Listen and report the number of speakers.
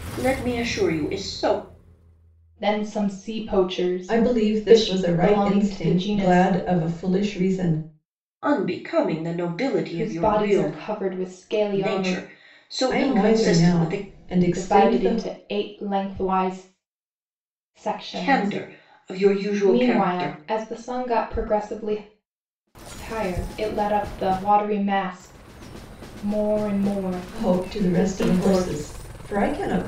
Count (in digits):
3